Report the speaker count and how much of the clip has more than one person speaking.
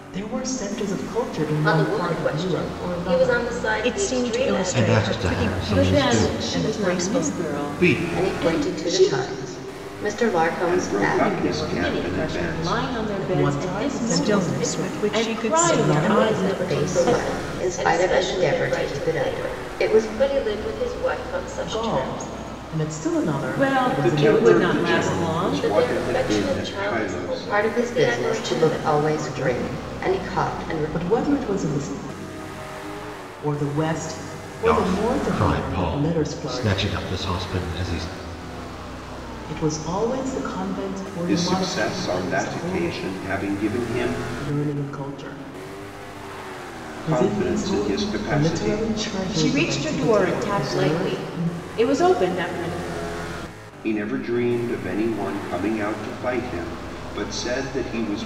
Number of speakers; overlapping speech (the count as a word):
seven, about 55%